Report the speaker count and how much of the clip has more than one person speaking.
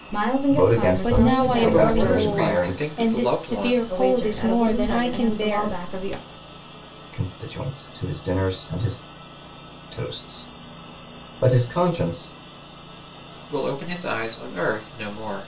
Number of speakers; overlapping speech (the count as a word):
four, about 34%